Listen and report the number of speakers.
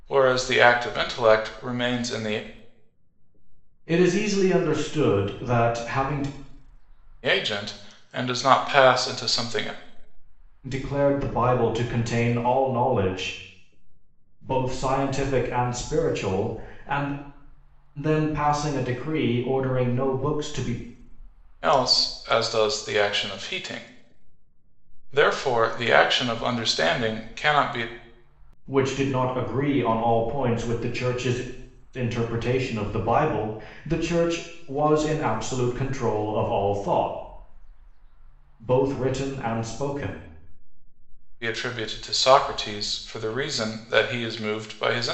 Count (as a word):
two